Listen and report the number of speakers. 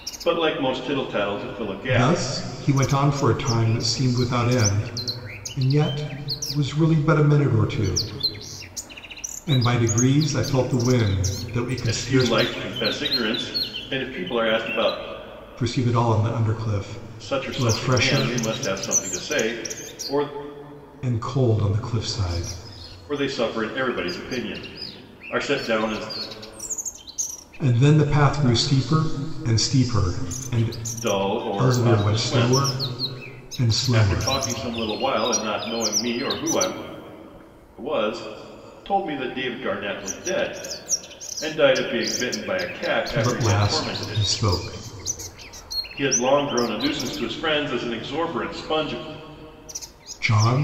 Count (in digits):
2